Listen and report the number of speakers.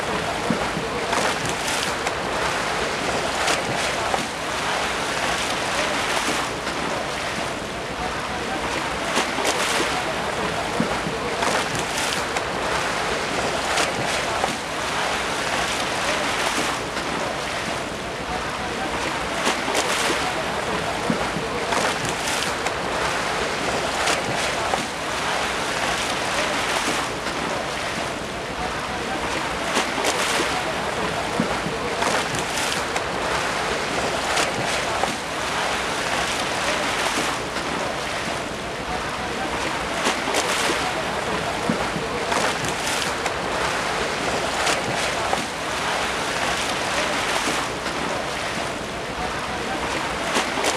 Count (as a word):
zero